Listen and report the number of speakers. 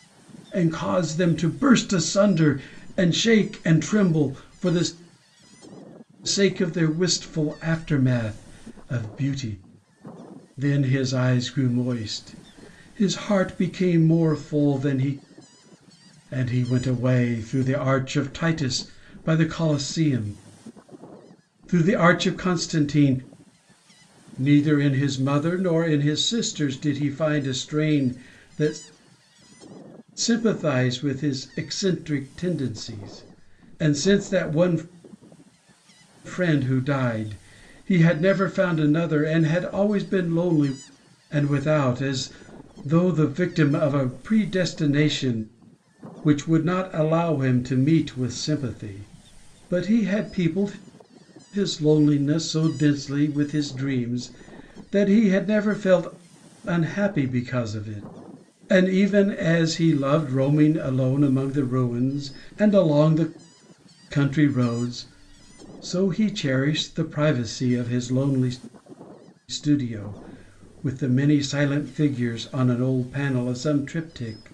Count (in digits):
1